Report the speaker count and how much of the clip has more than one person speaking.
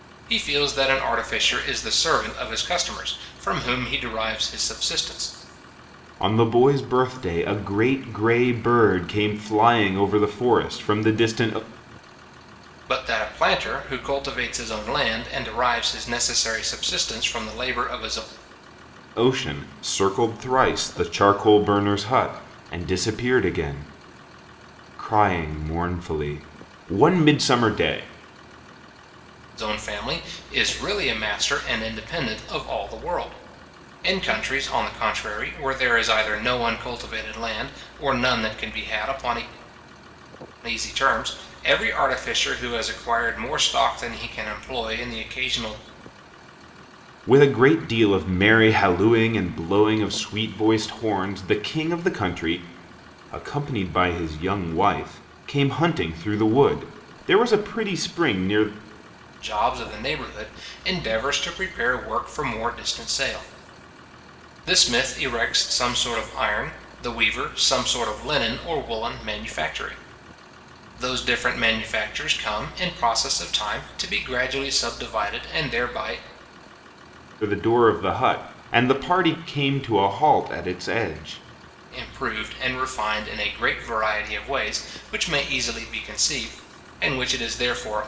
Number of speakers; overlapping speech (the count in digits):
2, no overlap